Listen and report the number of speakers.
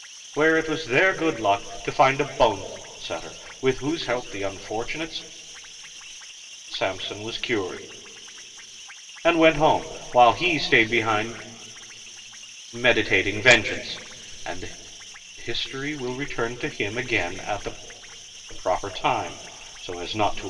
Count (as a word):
one